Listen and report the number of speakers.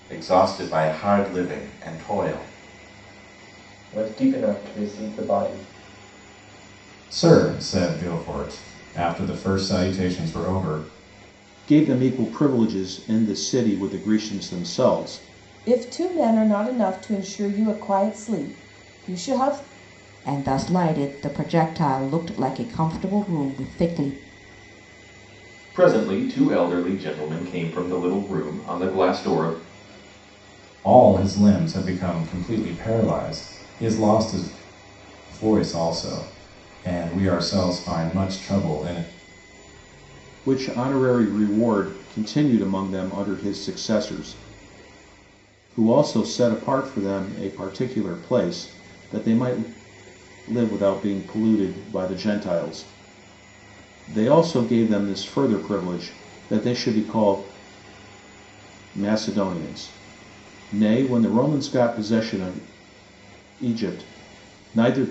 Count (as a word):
seven